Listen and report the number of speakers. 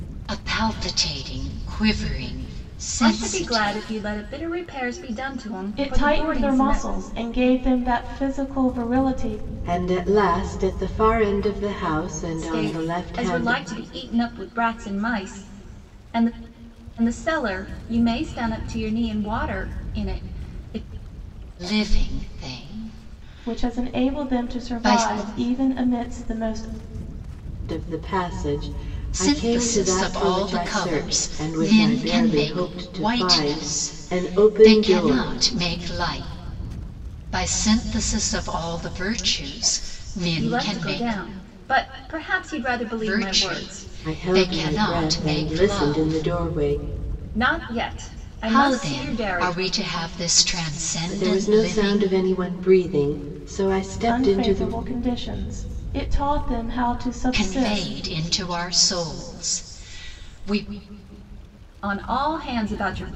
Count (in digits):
4